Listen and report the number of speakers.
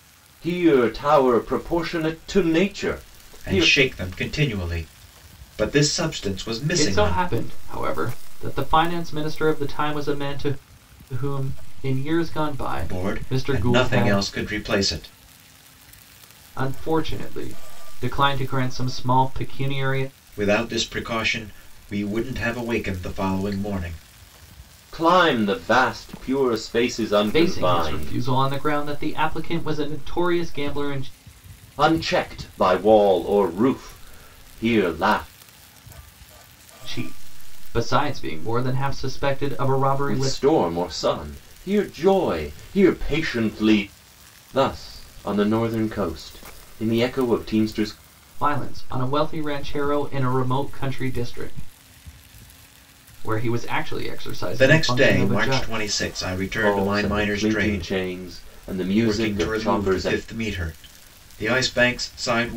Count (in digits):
3